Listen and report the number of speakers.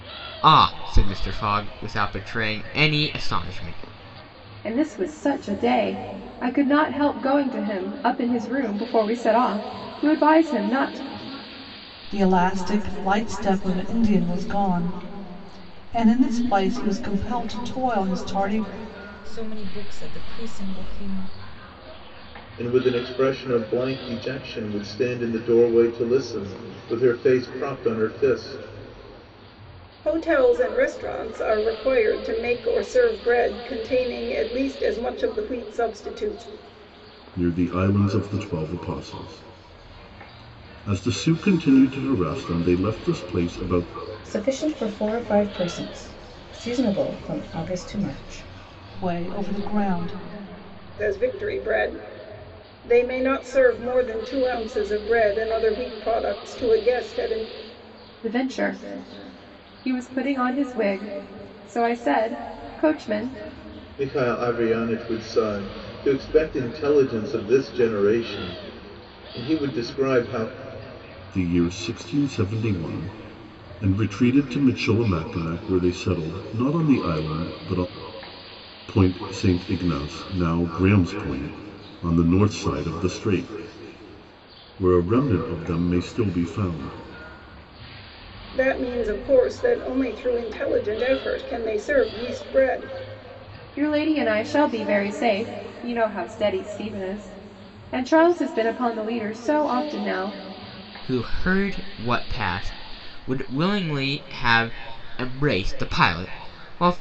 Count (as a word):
eight